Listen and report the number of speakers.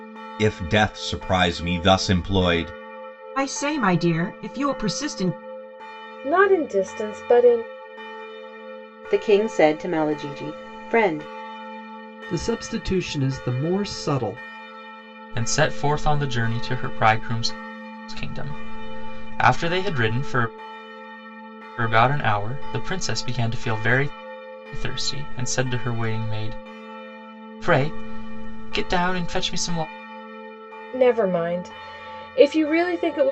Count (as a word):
six